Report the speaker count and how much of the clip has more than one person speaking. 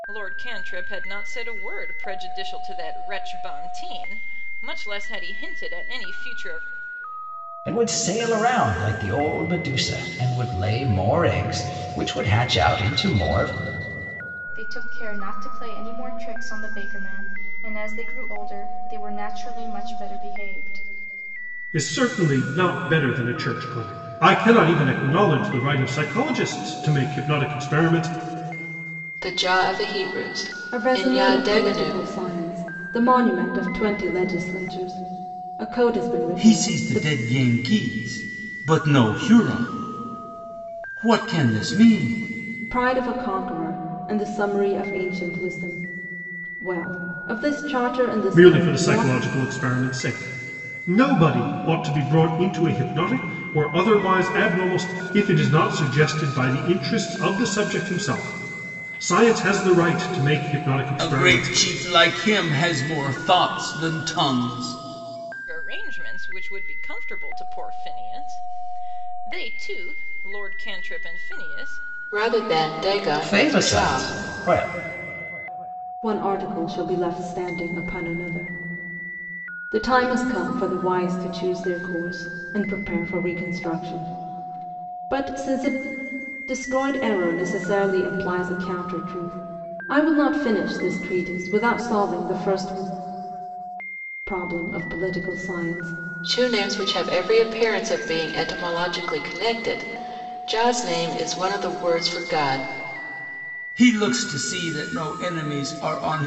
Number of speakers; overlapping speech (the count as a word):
seven, about 4%